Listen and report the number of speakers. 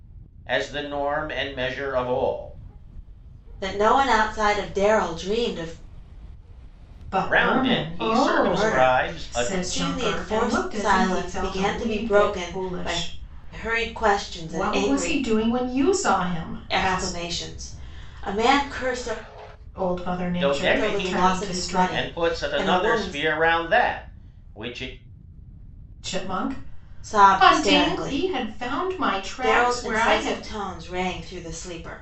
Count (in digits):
3